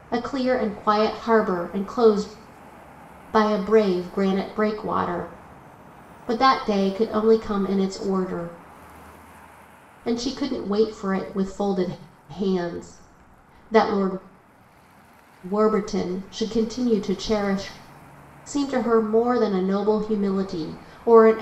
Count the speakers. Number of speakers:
1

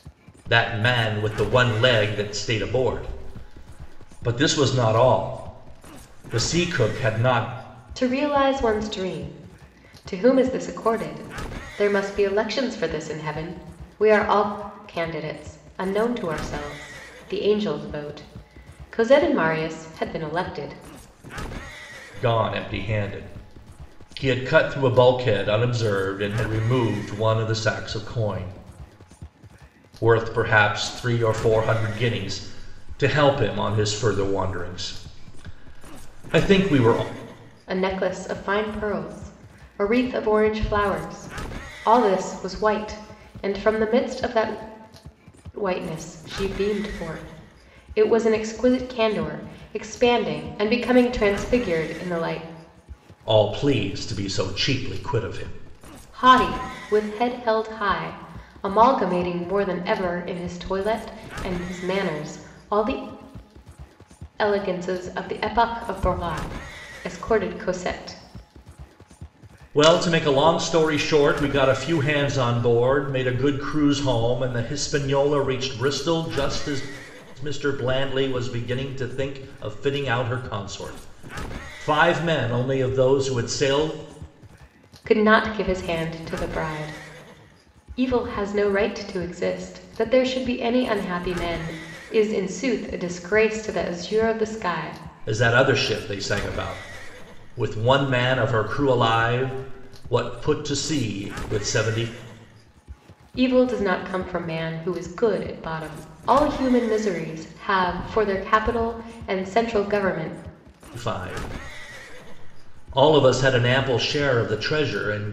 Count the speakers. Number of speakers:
2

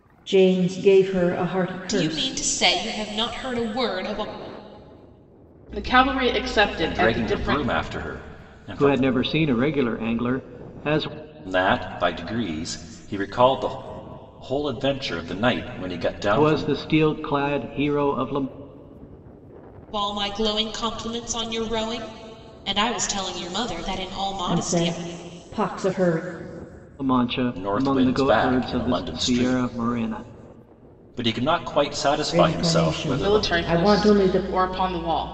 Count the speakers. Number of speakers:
5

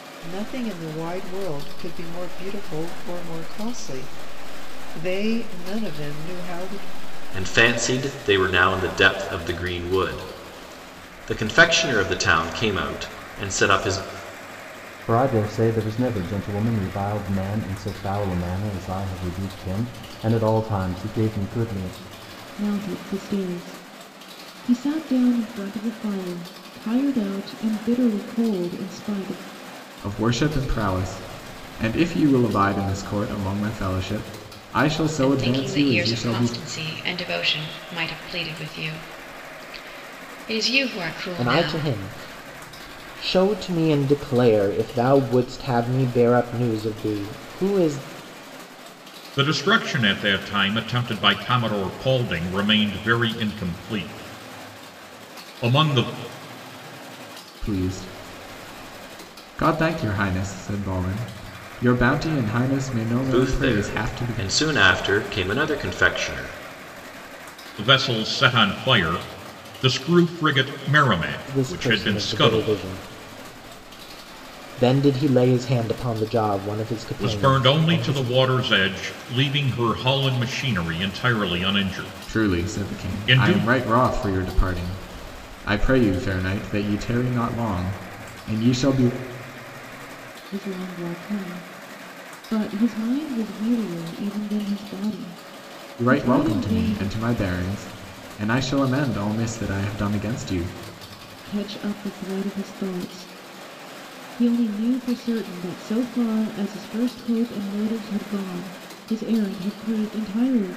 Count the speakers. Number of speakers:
8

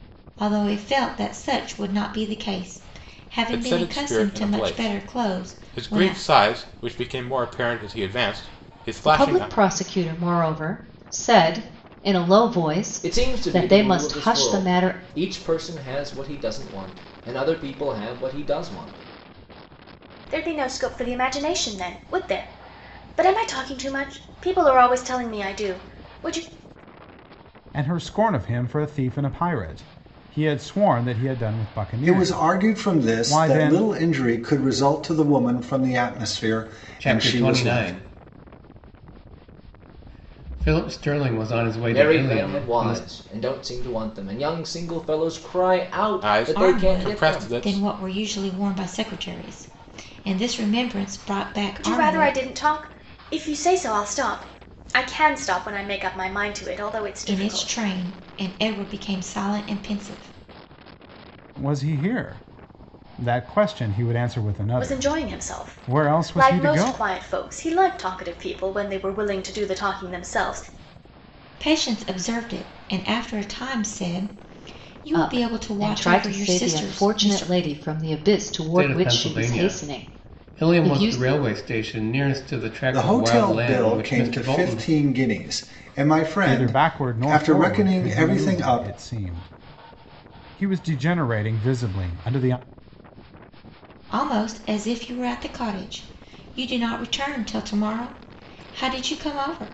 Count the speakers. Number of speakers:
8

